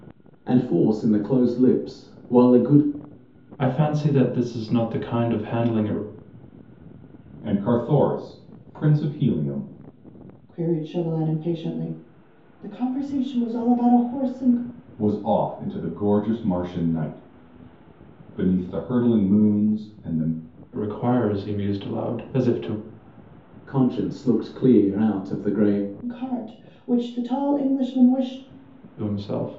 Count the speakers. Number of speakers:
4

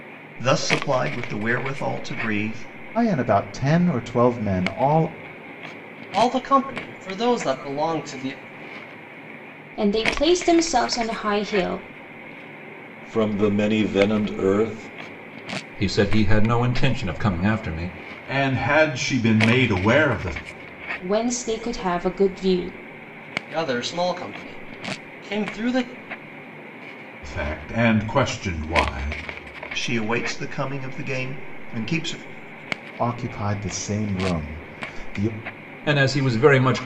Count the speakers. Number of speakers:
7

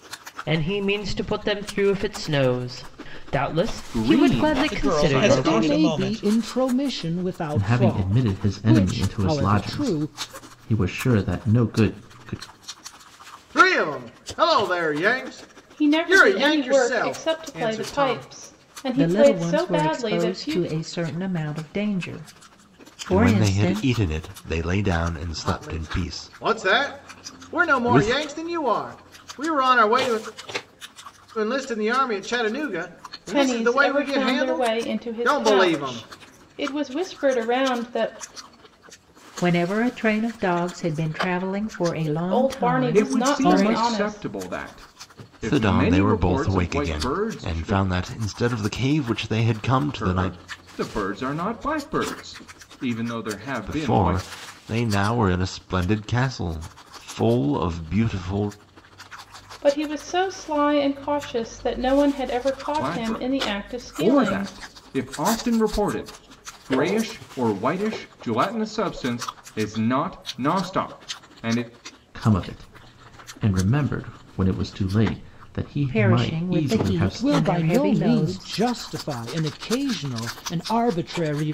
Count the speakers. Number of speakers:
9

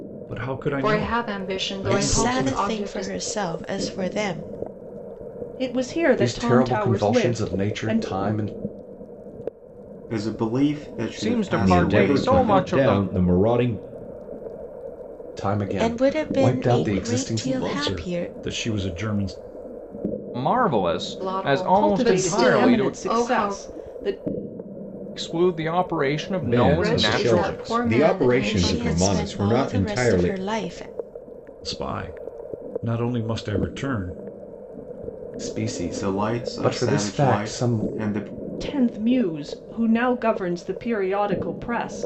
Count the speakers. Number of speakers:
8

